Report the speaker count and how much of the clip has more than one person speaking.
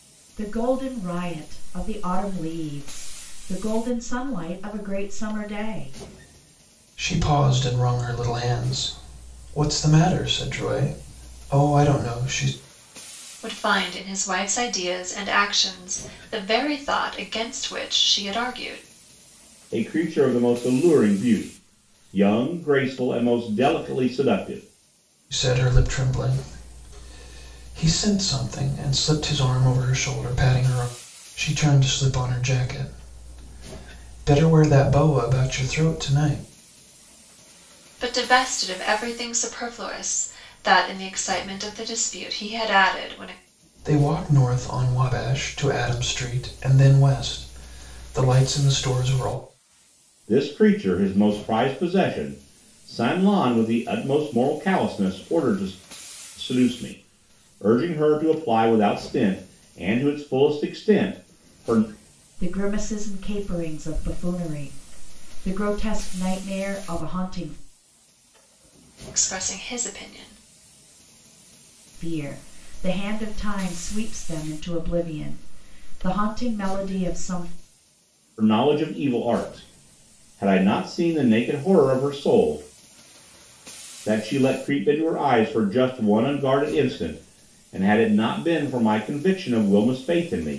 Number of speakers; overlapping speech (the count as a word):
four, no overlap